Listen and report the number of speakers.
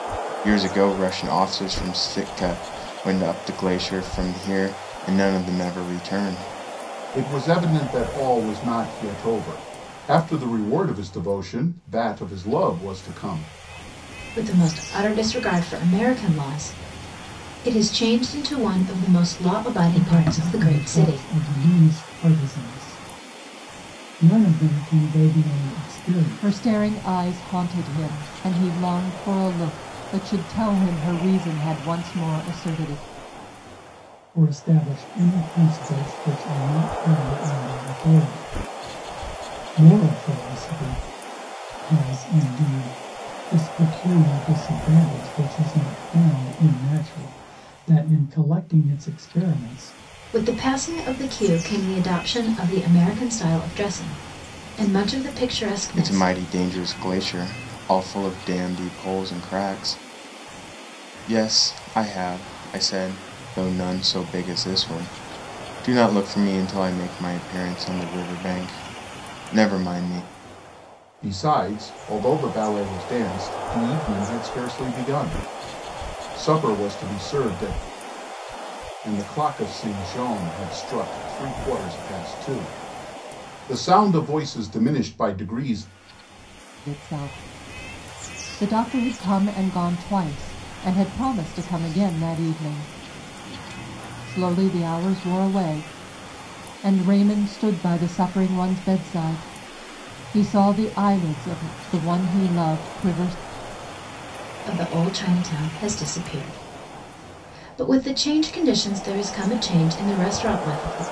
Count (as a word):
five